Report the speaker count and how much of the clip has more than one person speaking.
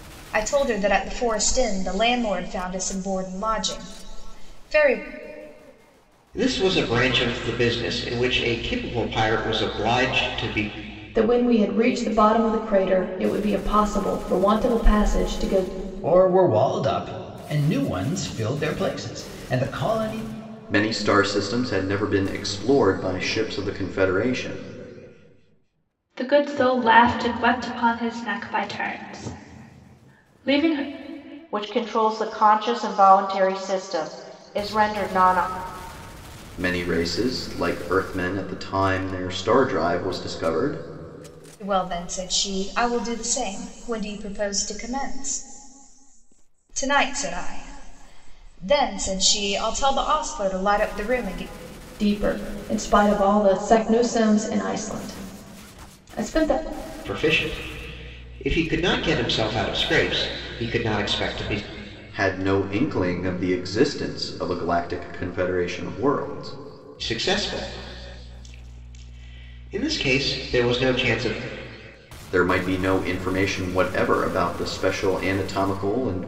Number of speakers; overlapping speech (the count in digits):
7, no overlap